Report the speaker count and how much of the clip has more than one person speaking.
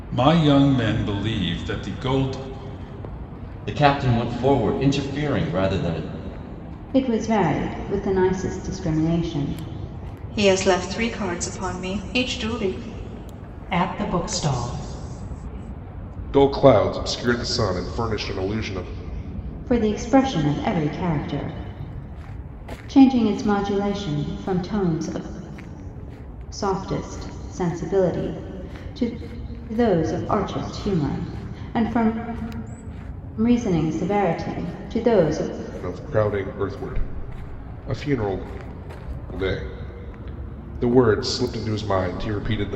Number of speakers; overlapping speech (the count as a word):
six, no overlap